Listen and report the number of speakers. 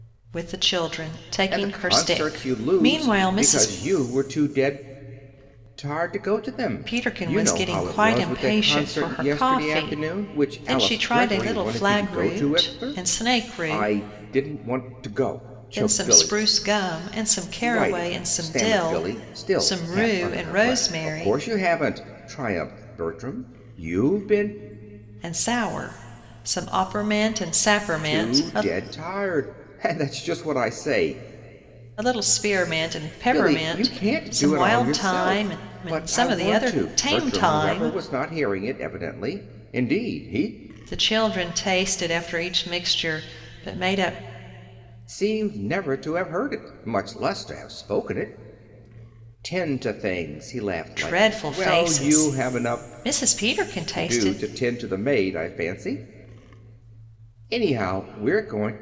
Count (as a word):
two